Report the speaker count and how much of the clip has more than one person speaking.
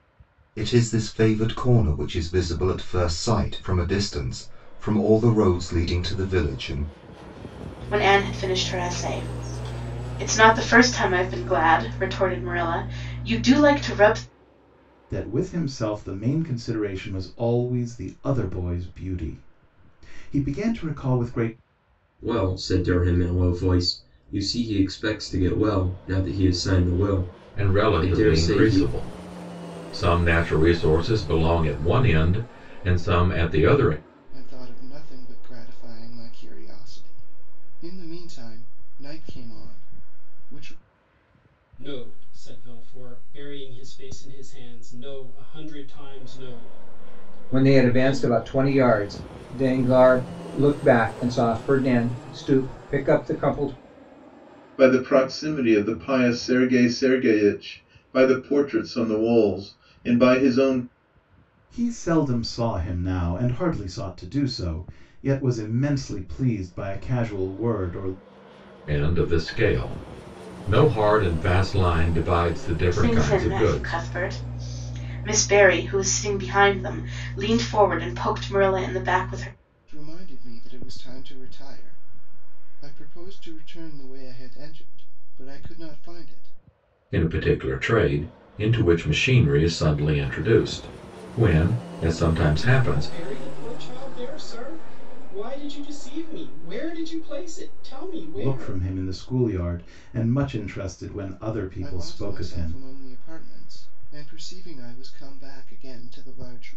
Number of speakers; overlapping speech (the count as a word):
nine, about 5%